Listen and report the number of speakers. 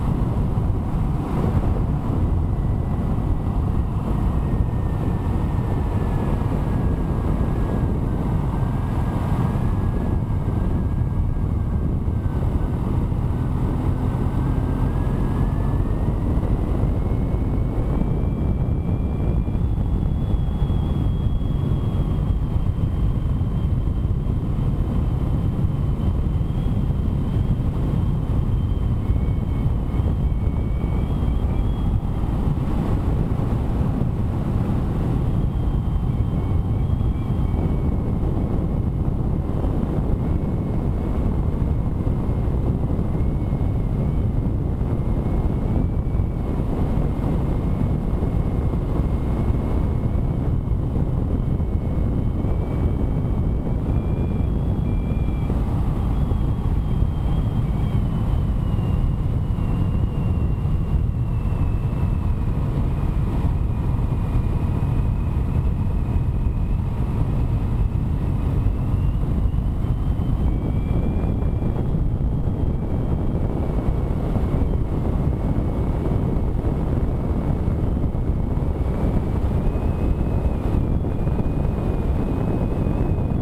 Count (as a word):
zero